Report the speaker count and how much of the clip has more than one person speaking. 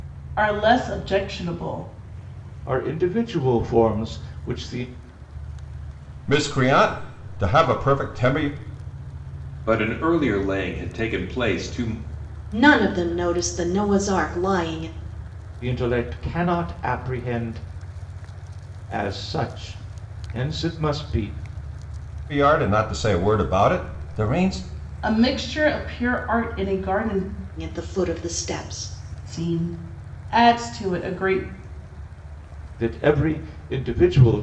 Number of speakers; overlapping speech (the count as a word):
five, no overlap